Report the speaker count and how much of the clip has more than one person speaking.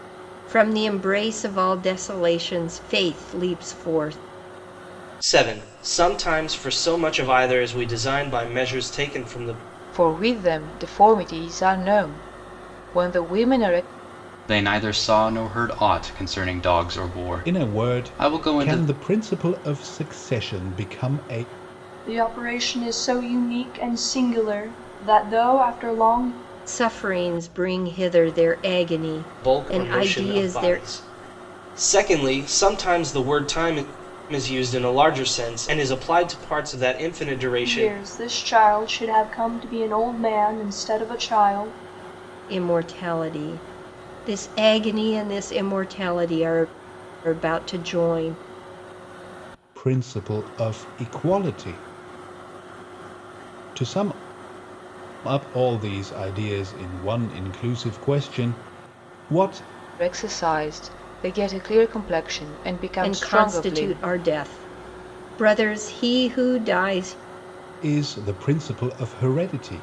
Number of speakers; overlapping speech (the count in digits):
6, about 6%